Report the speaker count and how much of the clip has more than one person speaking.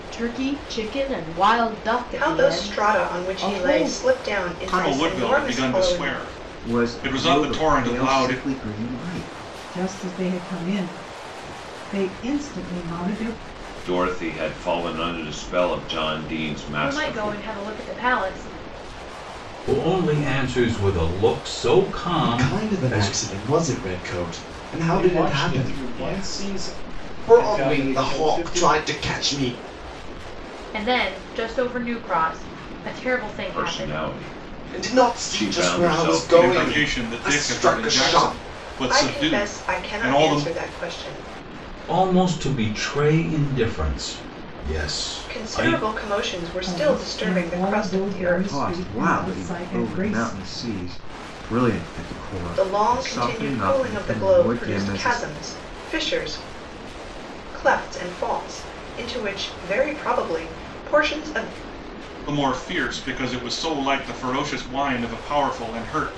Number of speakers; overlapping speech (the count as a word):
ten, about 37%